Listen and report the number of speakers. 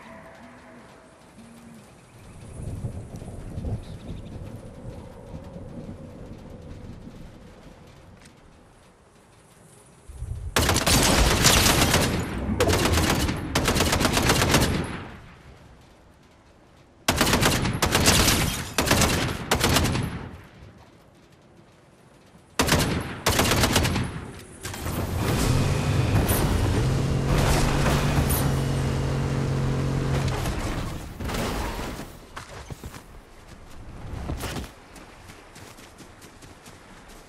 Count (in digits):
0